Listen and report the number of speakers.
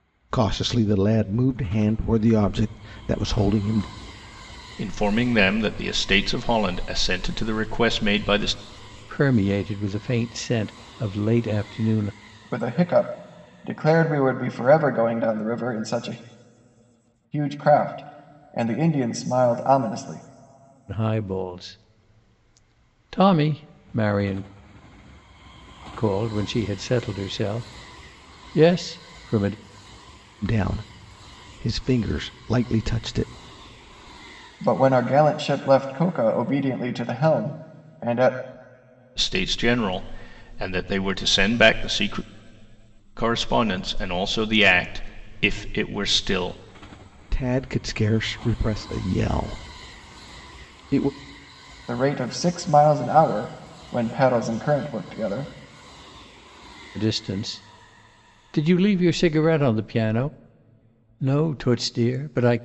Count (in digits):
4